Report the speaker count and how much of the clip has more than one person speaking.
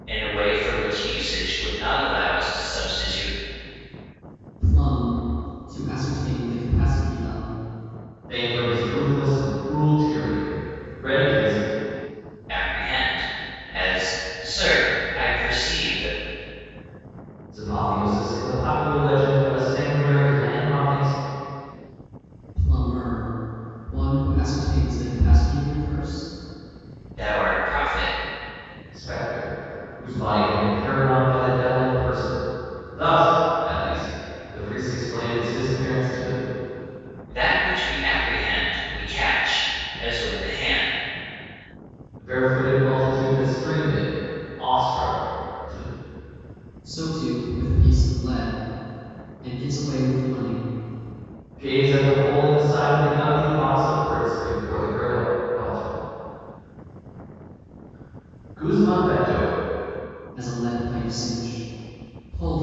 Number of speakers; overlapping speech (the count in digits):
3, no overlap